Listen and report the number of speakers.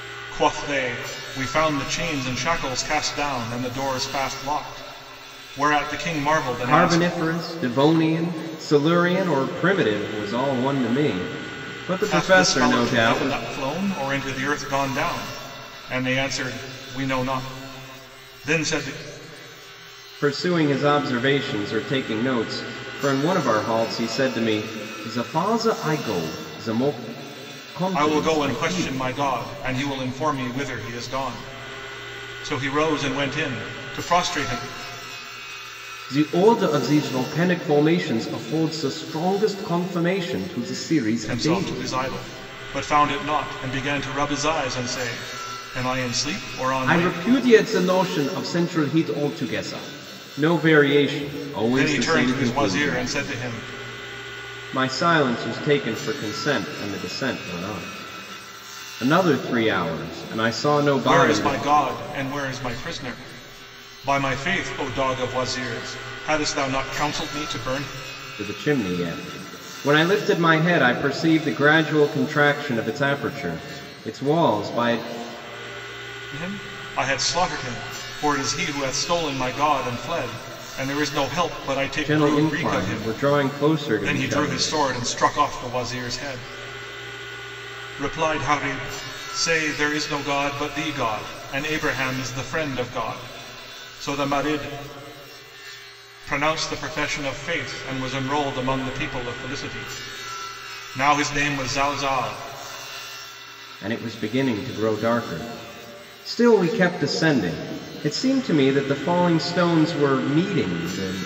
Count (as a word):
two